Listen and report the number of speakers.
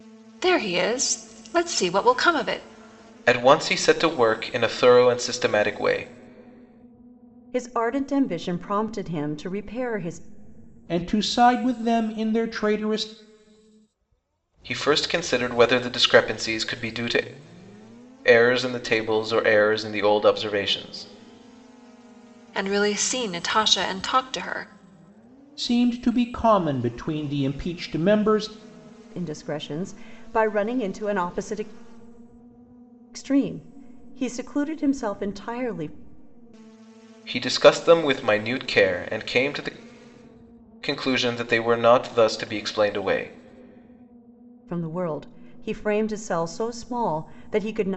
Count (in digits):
4